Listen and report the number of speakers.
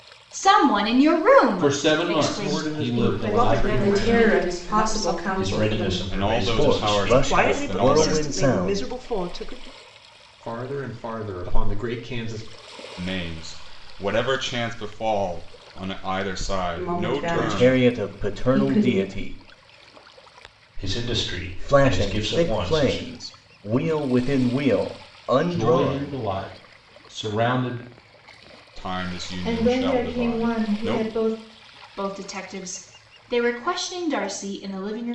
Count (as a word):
nine